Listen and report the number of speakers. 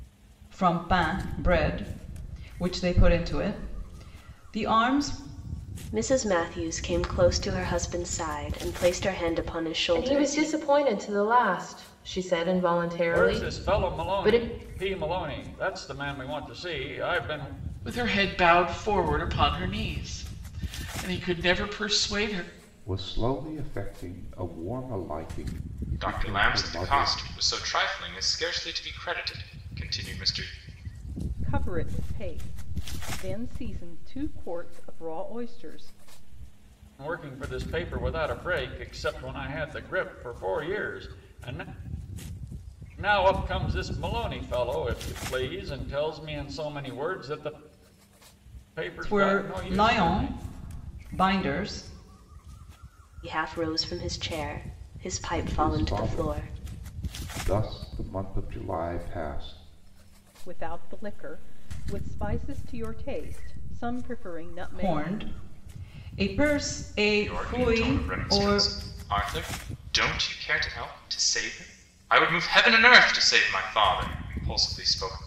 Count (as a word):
eight